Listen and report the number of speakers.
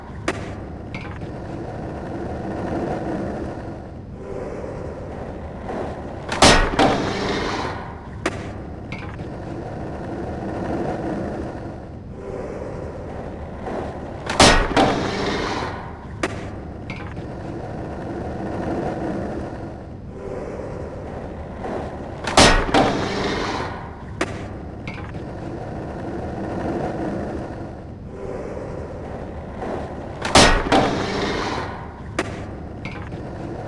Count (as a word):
zero